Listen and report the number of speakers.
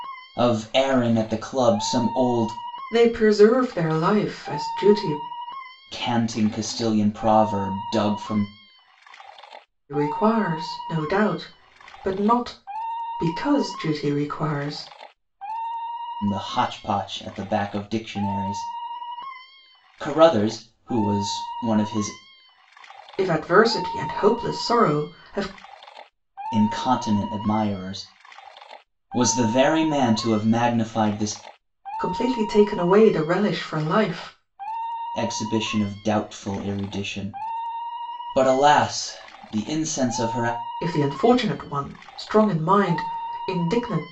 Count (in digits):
2